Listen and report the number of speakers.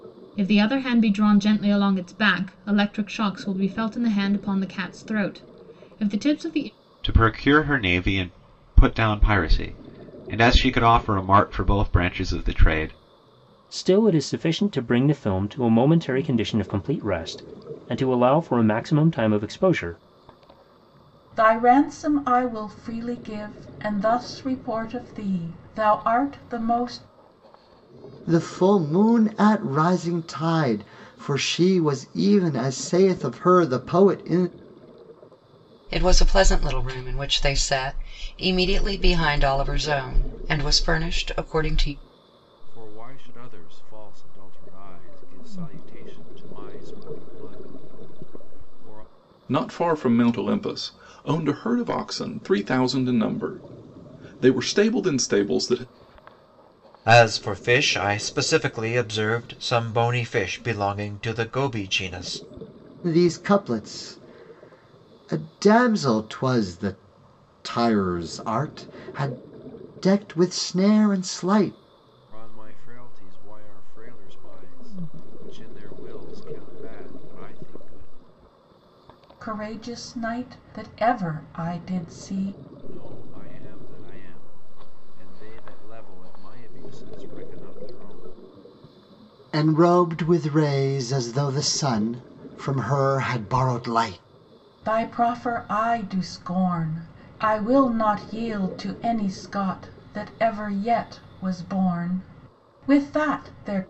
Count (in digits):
9